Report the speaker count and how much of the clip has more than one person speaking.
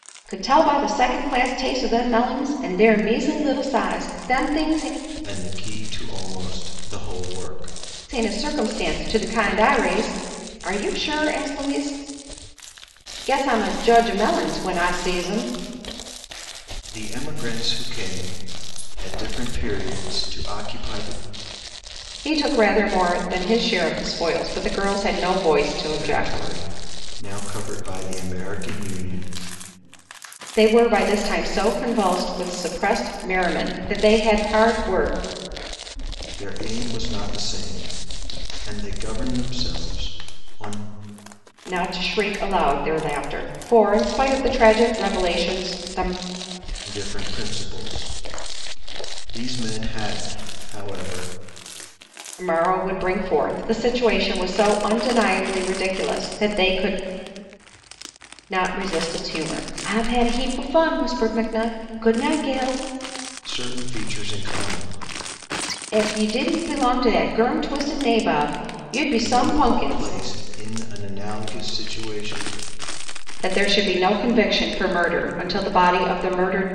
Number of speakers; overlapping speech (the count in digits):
2, about 3%